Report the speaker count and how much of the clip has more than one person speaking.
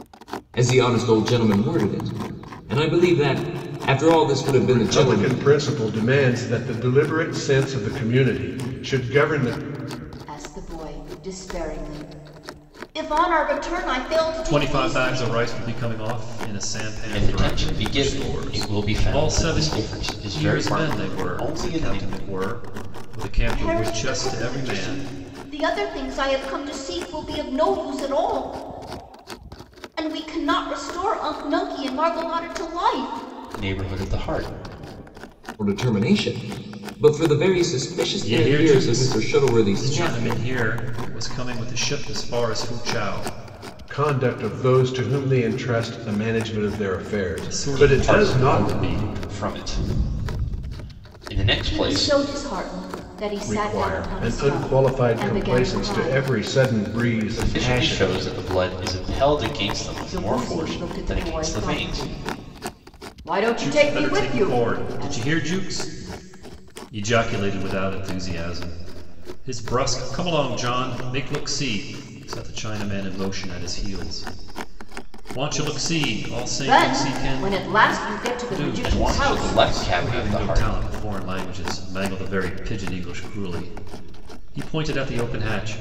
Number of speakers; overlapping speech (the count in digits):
5, about 28%